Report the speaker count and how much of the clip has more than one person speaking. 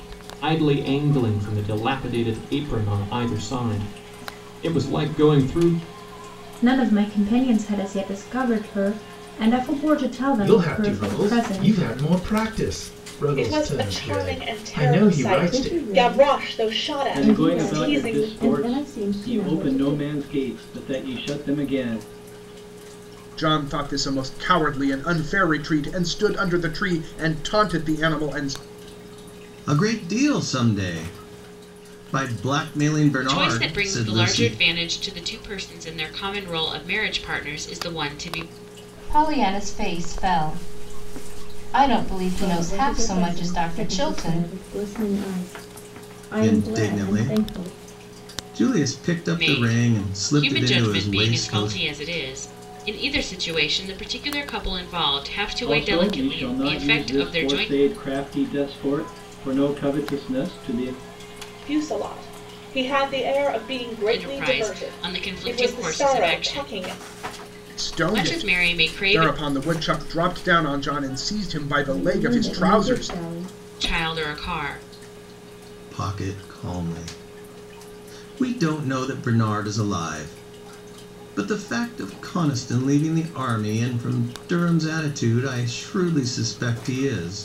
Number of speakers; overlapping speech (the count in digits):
10, about 27%